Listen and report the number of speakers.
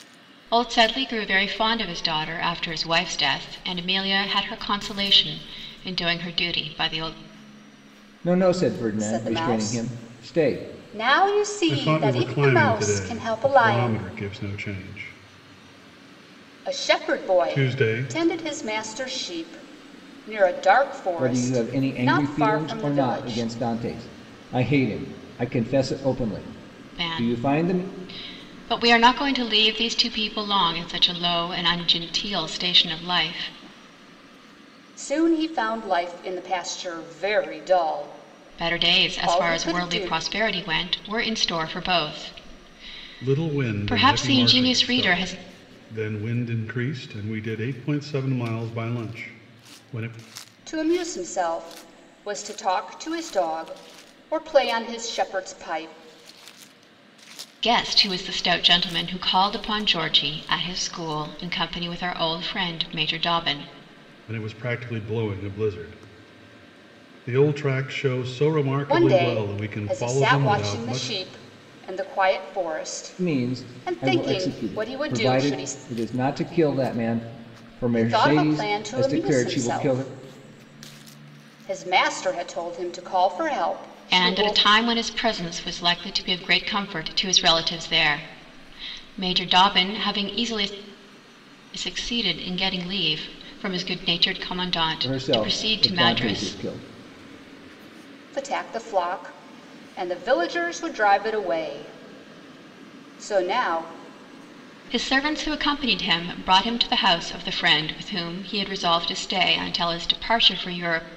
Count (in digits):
4